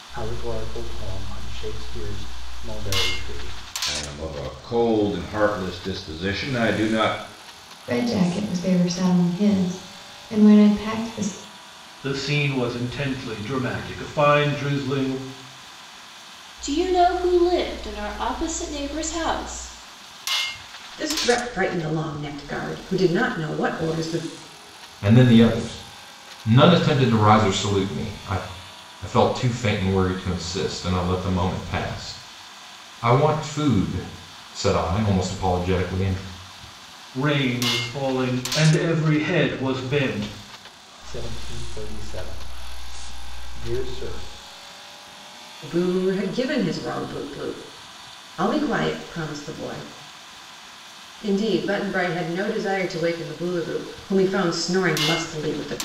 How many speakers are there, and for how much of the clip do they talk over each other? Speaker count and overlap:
7, no overlap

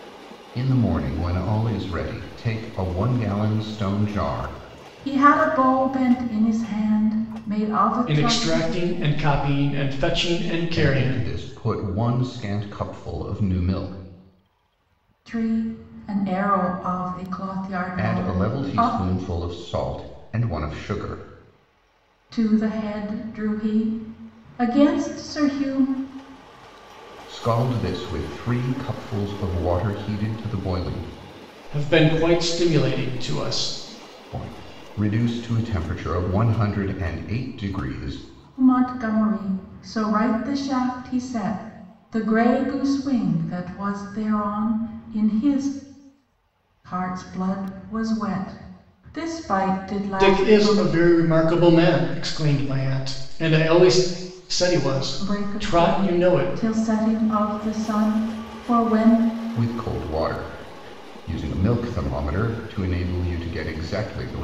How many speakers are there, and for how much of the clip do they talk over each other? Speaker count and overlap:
3, about 7%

